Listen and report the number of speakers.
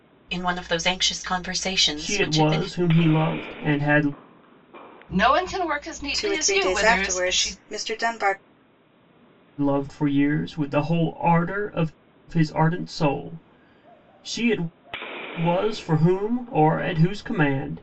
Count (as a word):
four